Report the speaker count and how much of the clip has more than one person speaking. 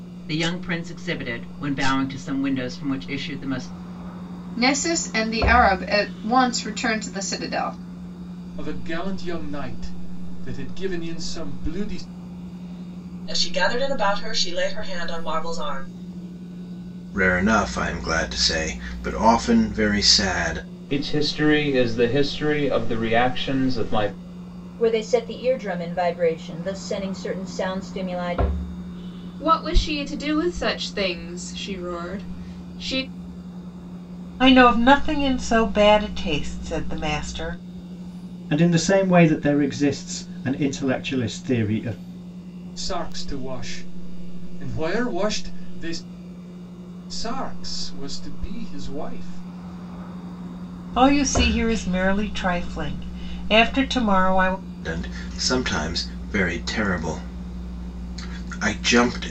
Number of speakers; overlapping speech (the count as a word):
ten, no overlap